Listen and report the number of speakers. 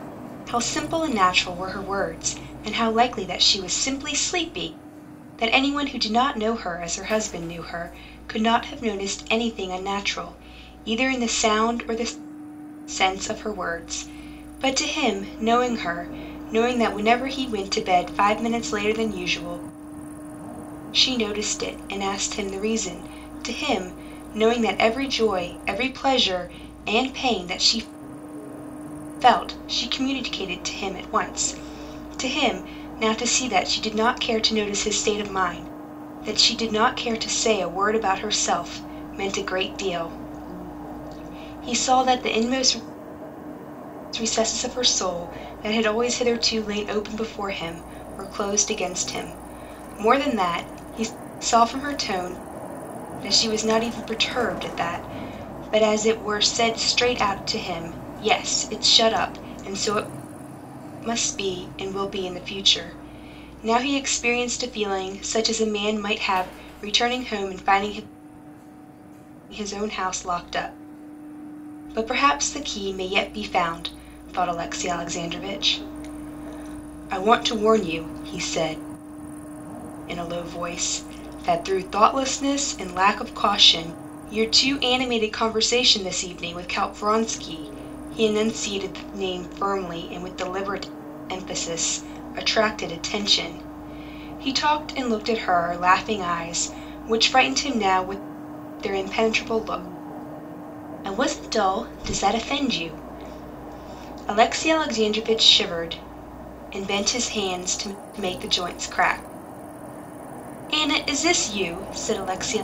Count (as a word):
one